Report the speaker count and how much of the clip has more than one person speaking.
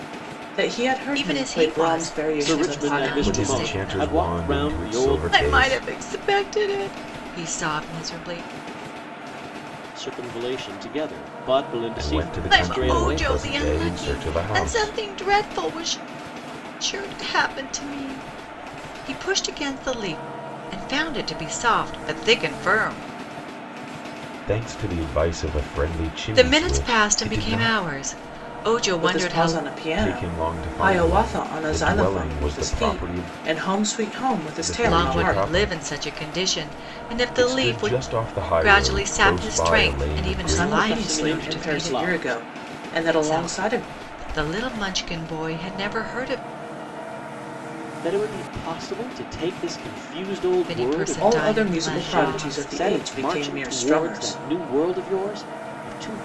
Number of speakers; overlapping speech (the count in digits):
4, about 42%